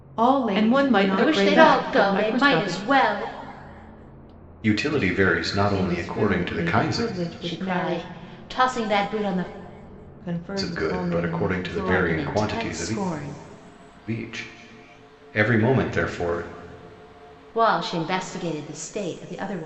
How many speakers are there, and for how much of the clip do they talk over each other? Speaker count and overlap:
4, about 35%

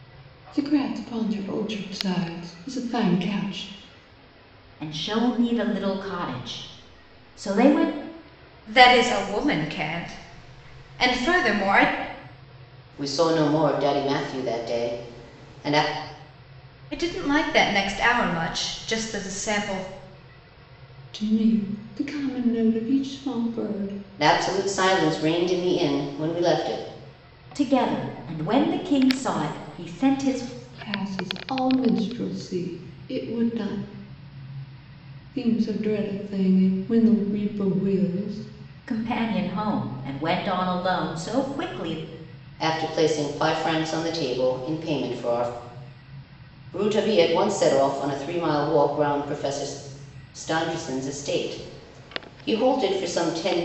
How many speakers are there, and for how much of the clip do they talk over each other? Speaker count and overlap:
4, no overlap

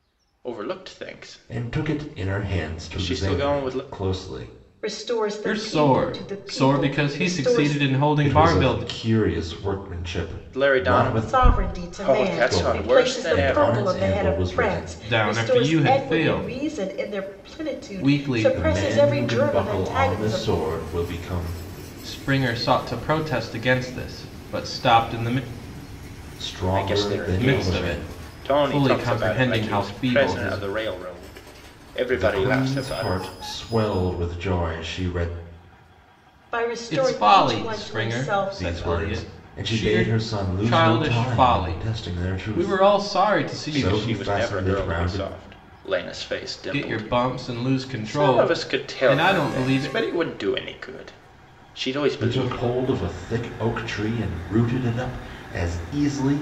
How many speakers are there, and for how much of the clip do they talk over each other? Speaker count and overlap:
4, about 57%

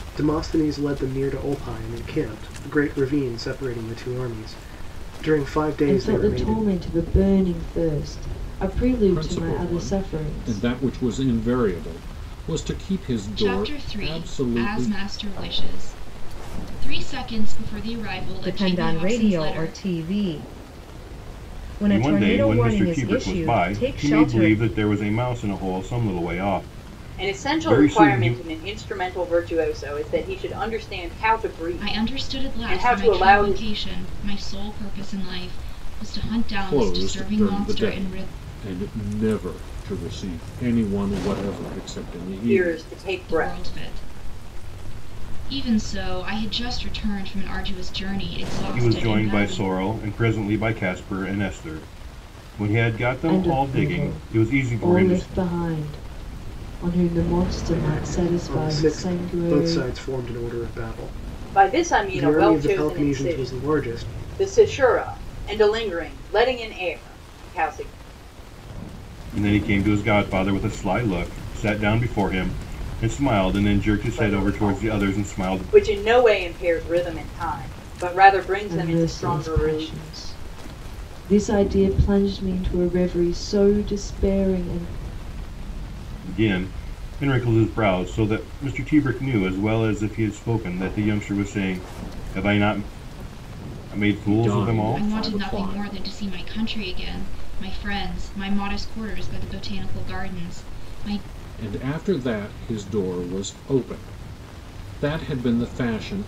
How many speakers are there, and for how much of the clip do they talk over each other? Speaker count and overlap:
7, about 25%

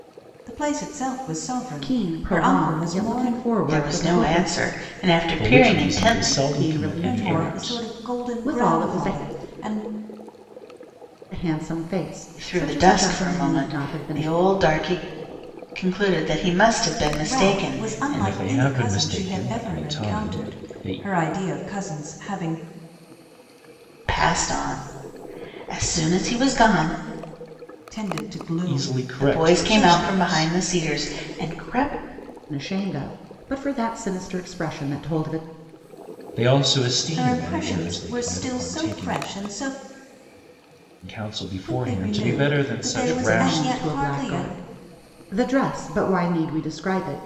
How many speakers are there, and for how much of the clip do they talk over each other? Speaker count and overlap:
4, about 40%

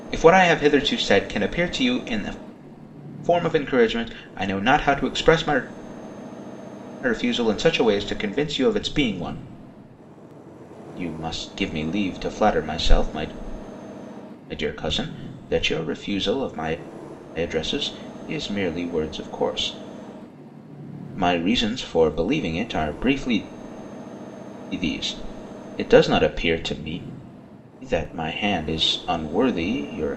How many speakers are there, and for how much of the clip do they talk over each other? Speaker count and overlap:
1, no overlap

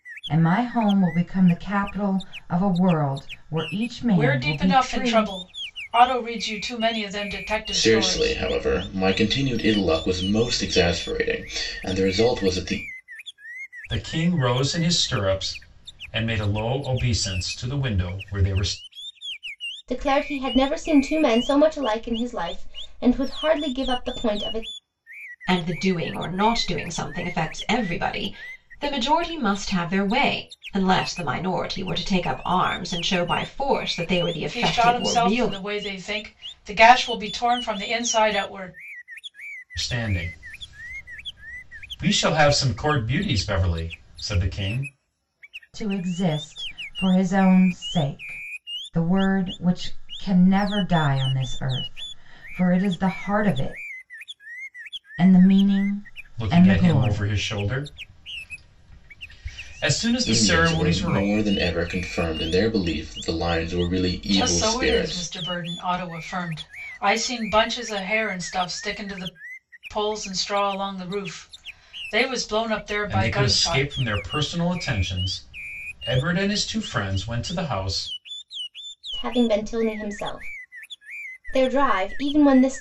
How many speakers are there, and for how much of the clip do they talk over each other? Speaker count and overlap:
6, about 8%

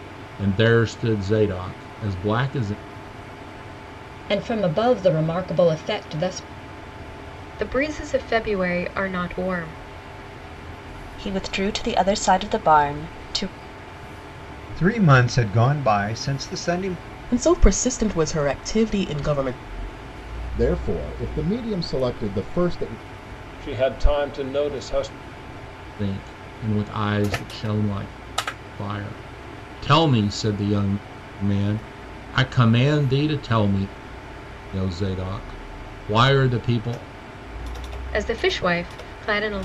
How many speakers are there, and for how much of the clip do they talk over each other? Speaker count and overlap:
8, no overlap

